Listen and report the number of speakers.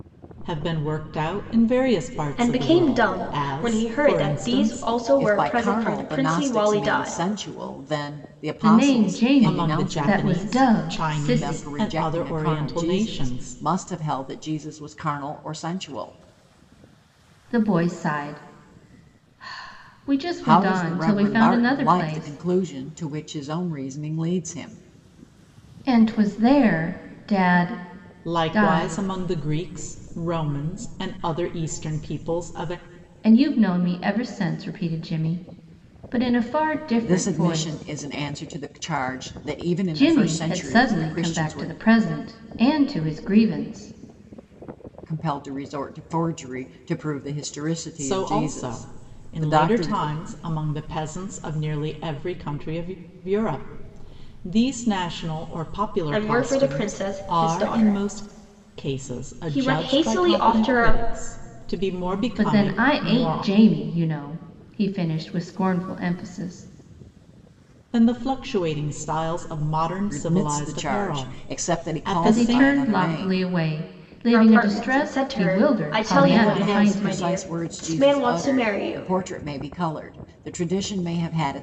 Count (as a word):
four